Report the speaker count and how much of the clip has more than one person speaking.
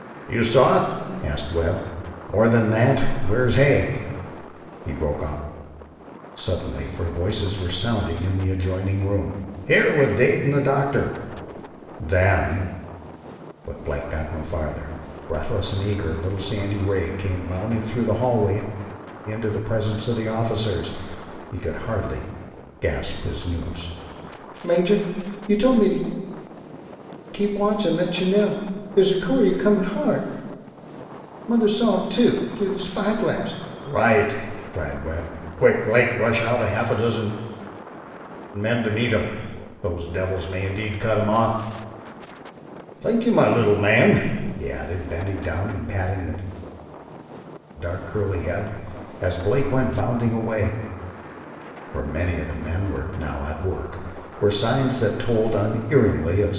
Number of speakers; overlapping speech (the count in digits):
1, no overlap